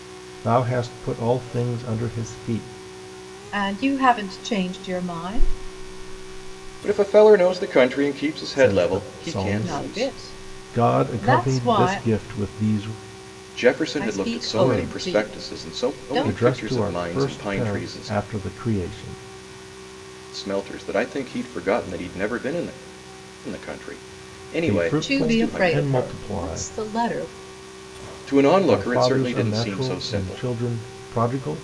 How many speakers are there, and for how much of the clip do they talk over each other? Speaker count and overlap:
three, about 35%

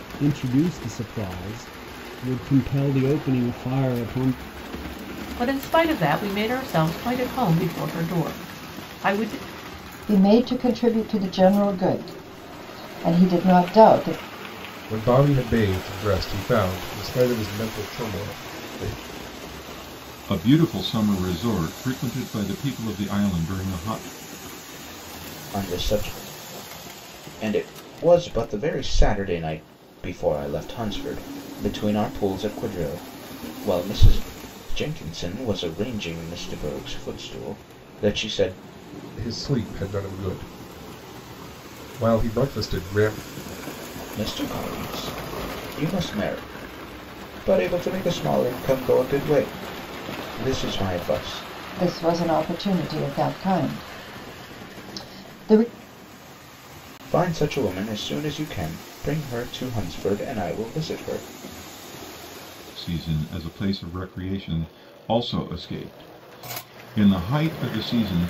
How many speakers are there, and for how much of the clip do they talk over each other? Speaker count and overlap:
six, no overlap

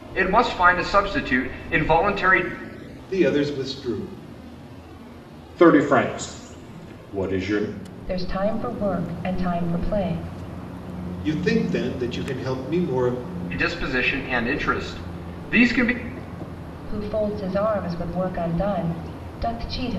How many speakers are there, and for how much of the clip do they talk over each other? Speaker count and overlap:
four, no overlap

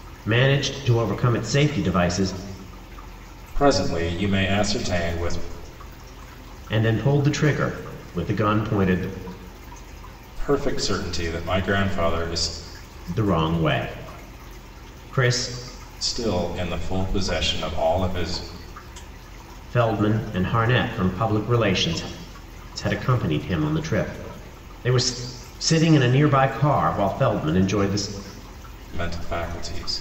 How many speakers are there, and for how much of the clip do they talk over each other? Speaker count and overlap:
two, no overlap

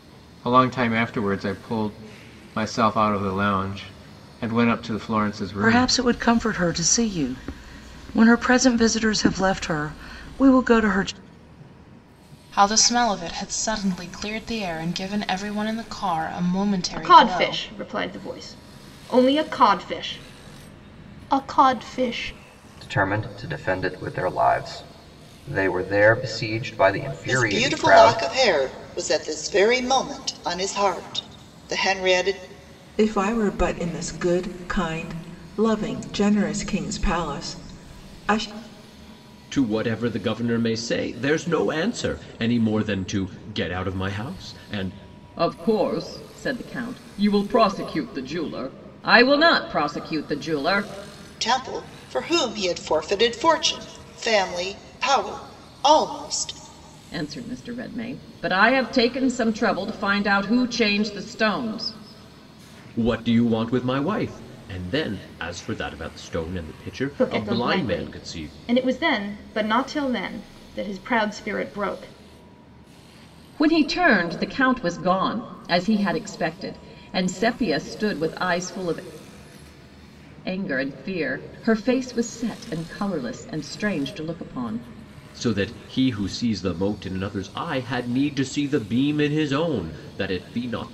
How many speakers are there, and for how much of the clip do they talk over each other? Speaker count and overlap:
nine, about 4%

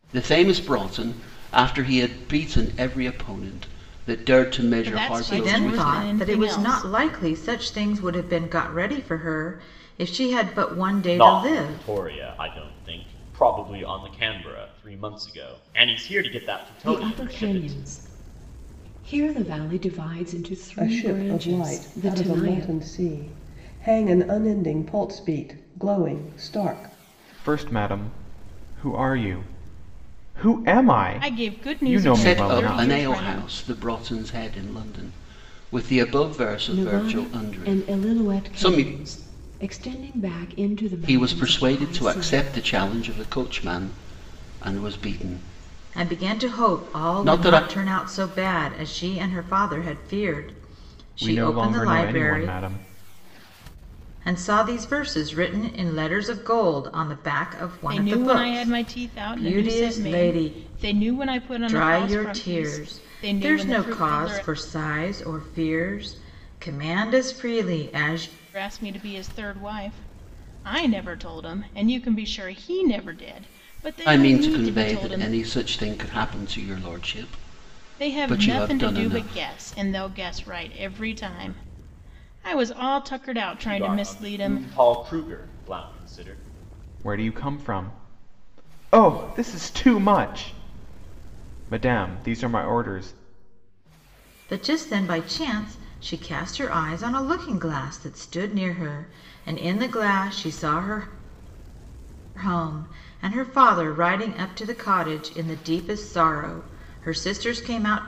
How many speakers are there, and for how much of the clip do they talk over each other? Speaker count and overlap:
seven, about 23%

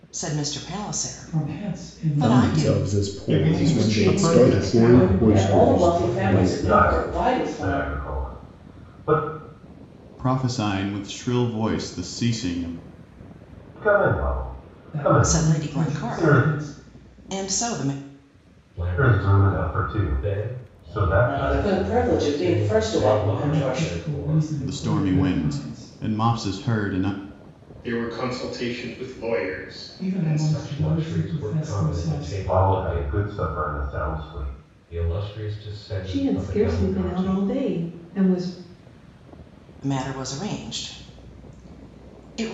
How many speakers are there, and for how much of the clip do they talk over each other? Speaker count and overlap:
ten, about 47%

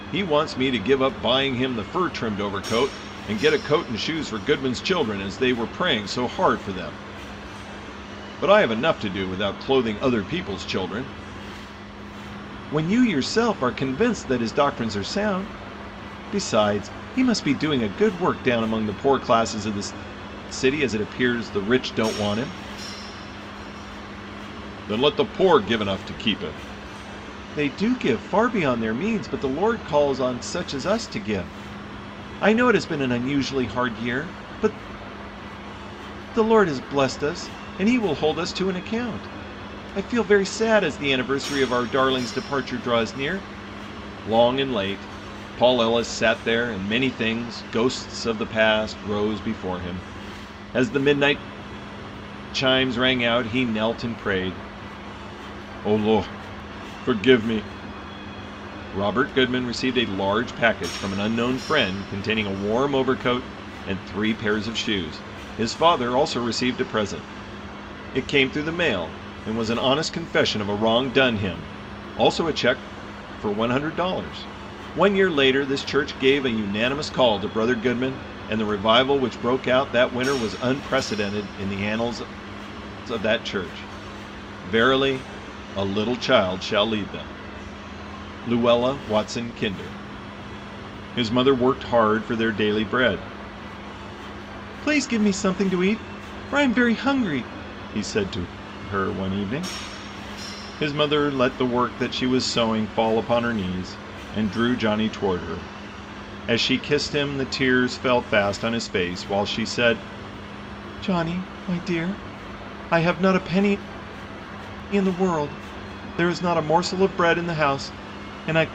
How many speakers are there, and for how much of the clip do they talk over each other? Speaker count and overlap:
one, no overlap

